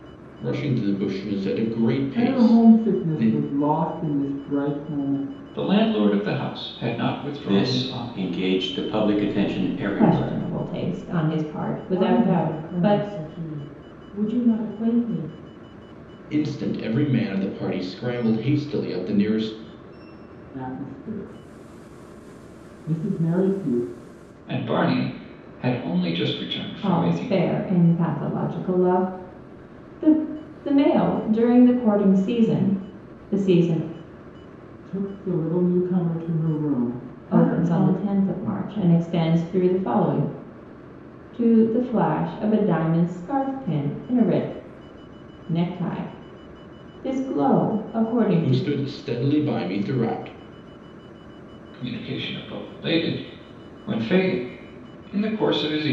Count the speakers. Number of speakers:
six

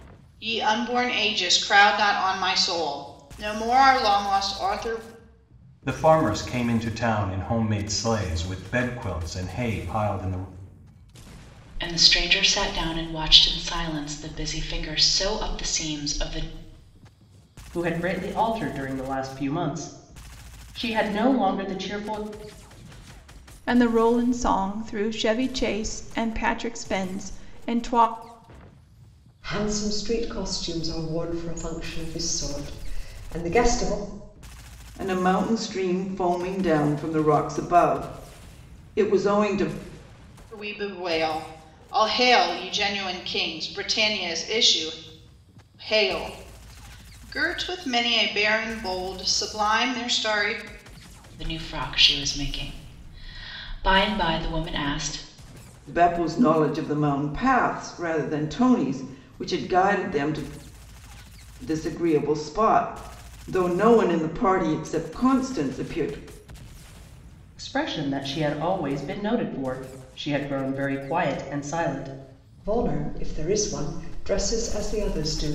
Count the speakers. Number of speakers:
seven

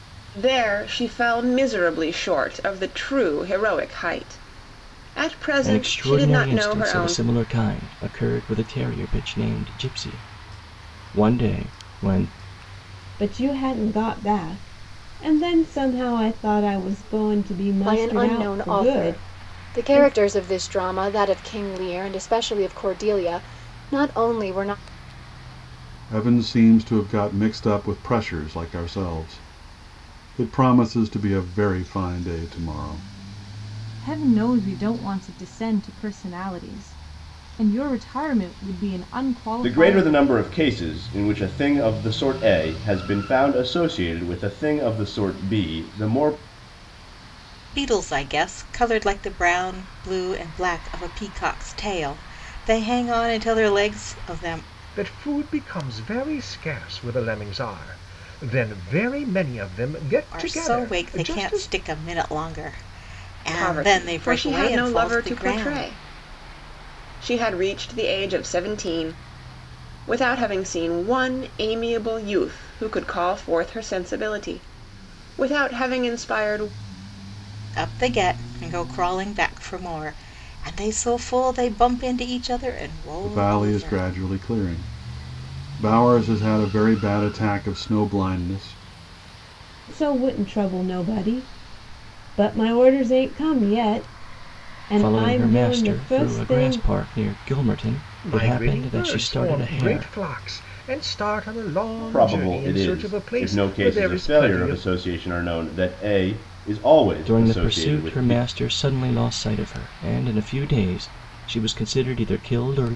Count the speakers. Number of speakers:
nine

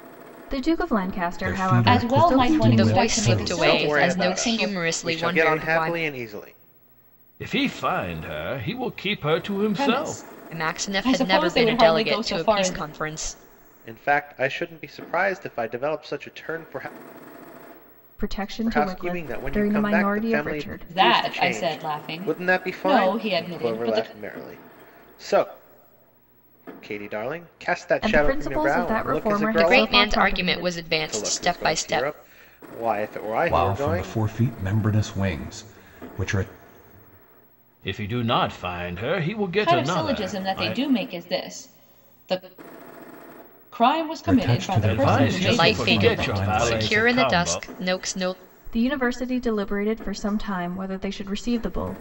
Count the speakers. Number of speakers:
six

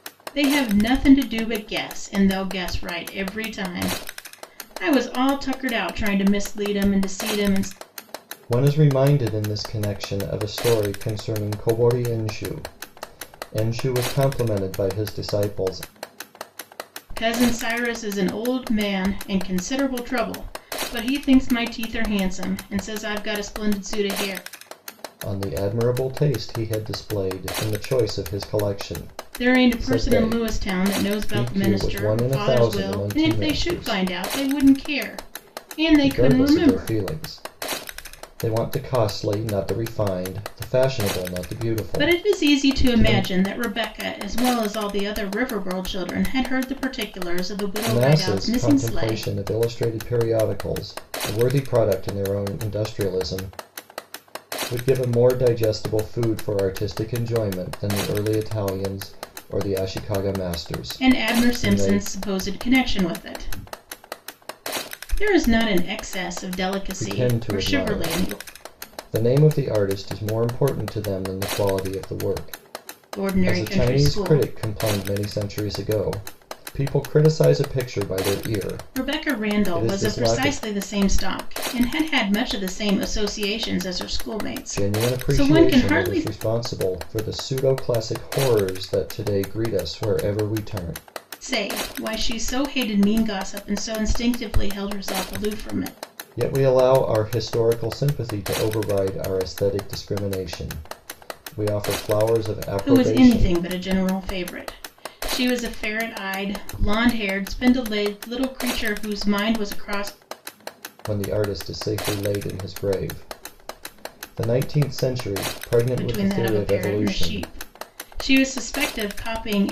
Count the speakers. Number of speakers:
two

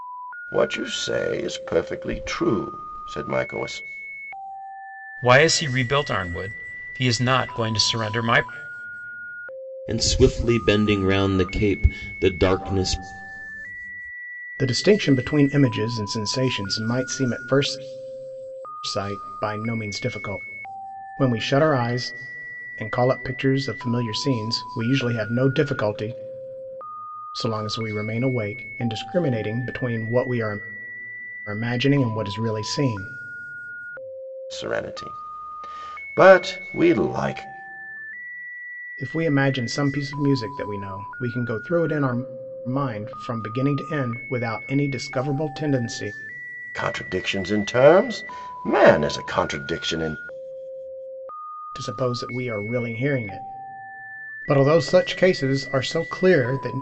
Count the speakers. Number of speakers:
four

